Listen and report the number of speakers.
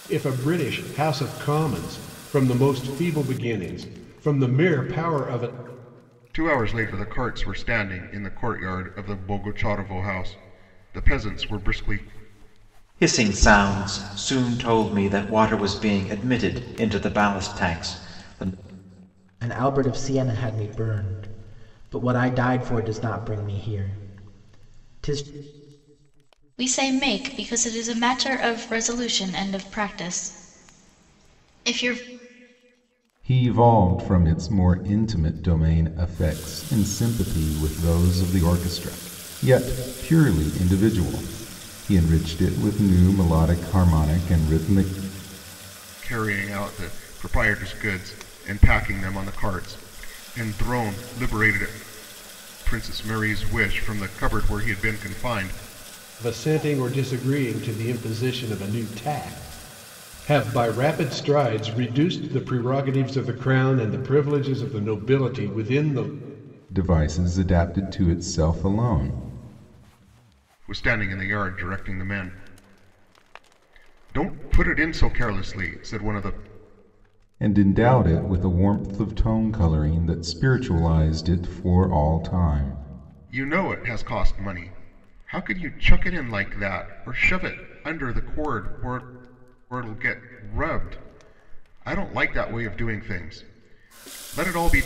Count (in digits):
6